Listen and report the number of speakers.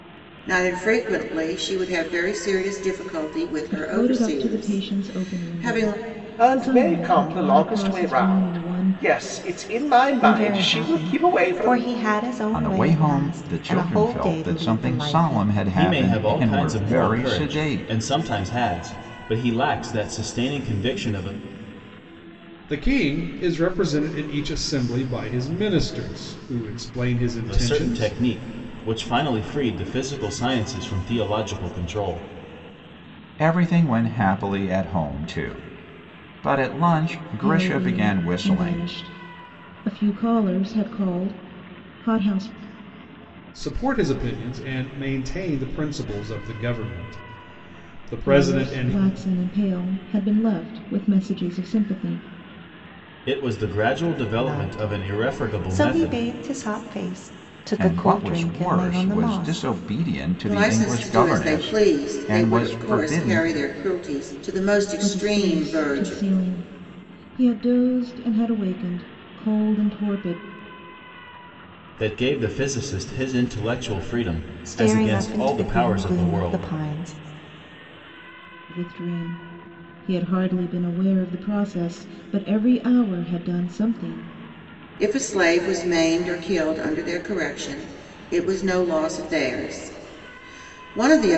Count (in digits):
7